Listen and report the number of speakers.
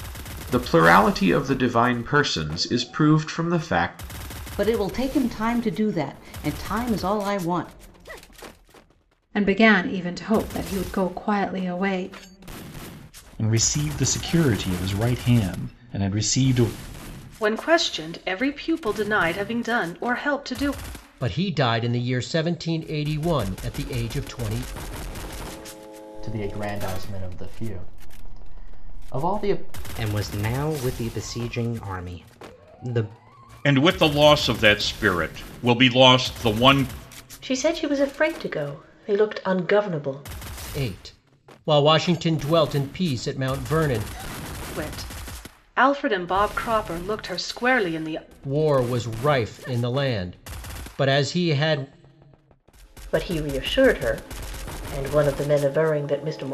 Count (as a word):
ten